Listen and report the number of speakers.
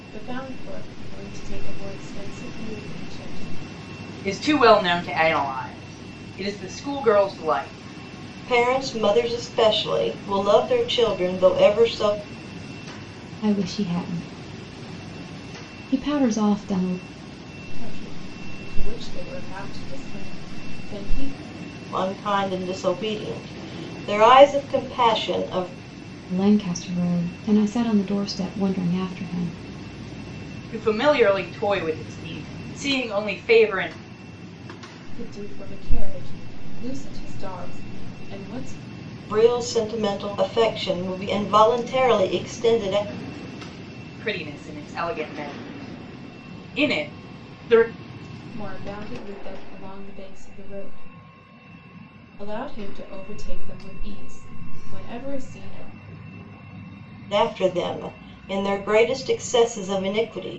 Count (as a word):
four